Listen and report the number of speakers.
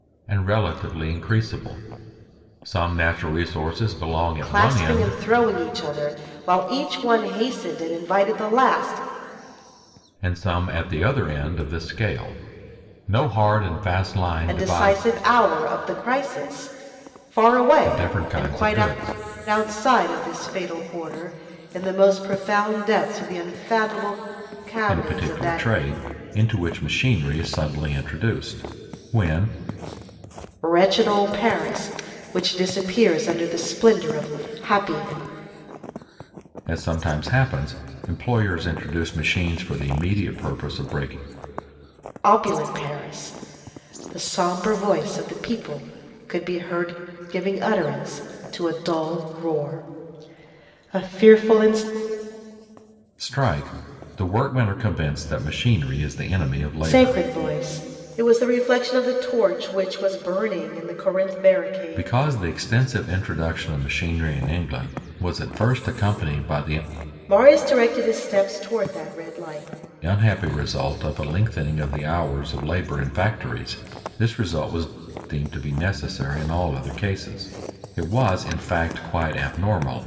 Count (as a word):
two